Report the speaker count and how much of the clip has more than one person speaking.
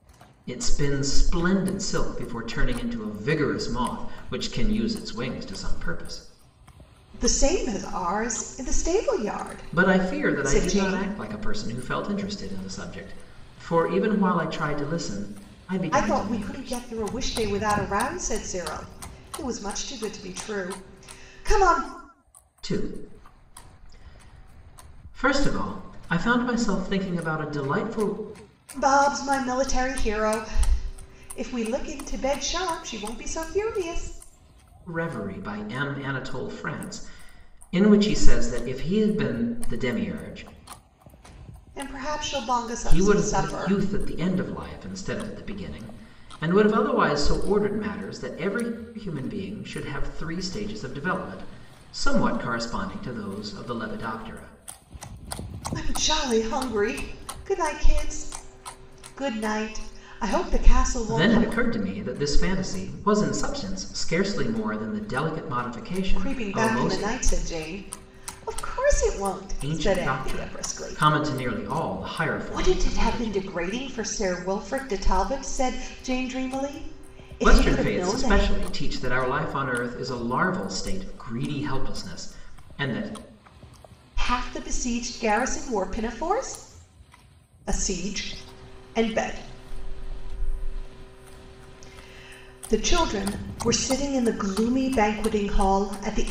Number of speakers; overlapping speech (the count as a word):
two, about 9%